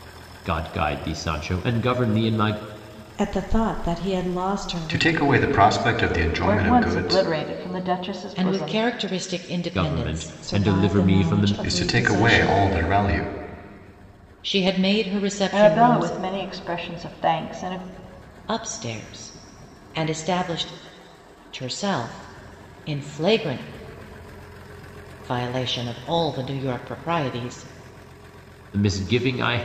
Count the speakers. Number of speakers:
five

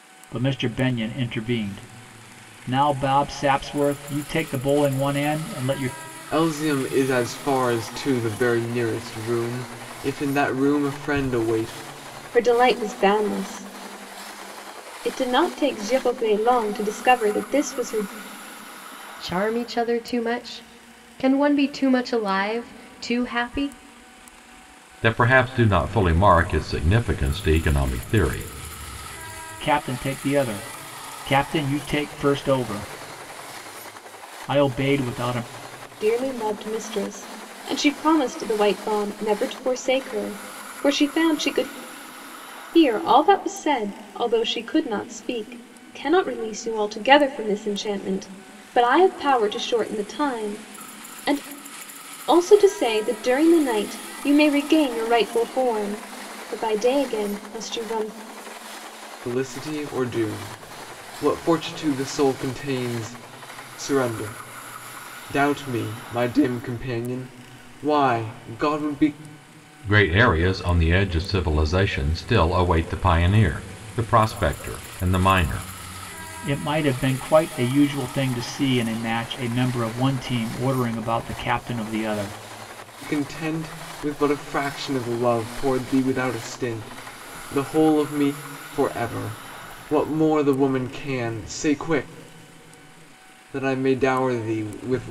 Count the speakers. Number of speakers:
five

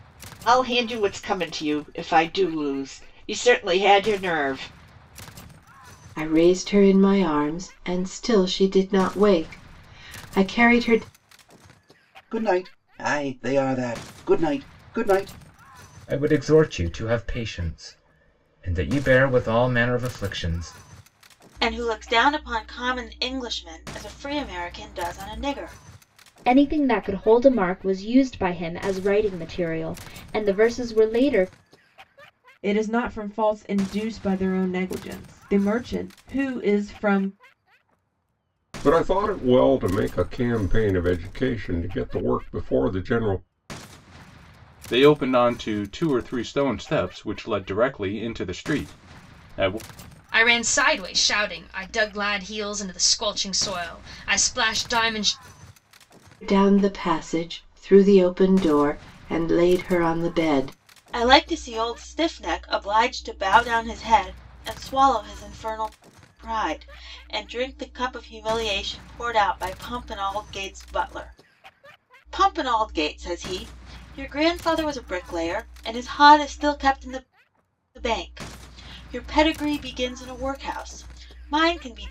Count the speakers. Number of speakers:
ten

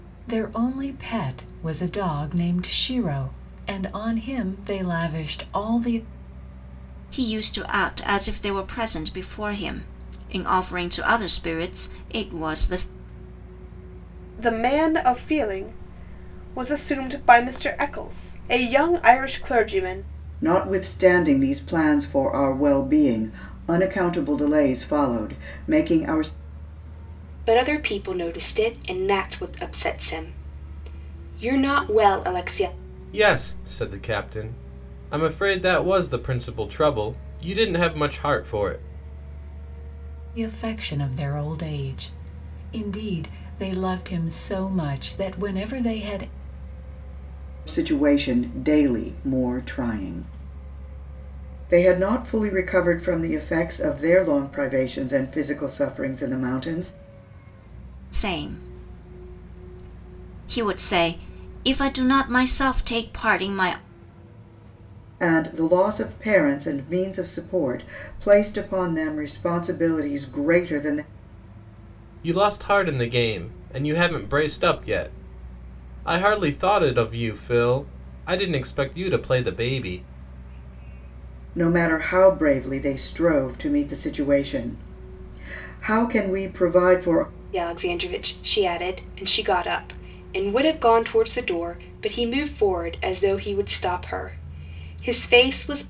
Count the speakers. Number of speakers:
six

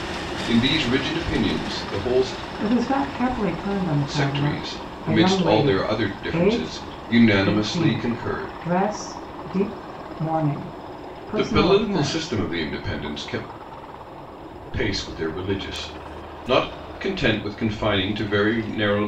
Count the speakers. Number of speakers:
two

